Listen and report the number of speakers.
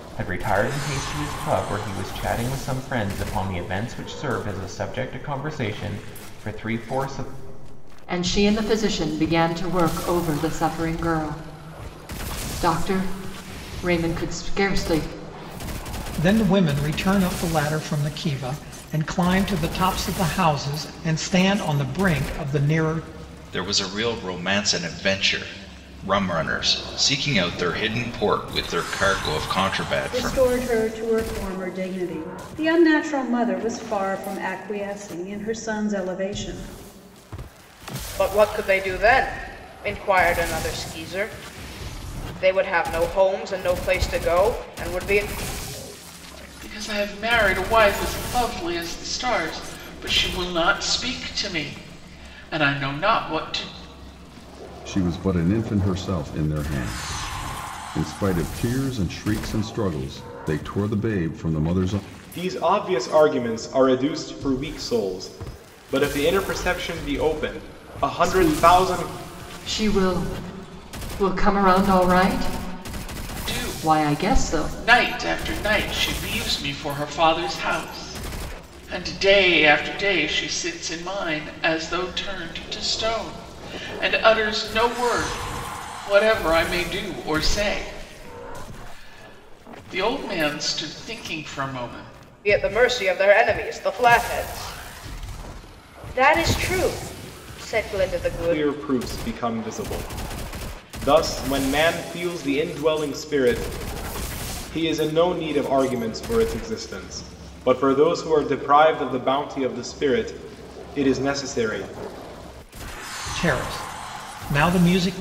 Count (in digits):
9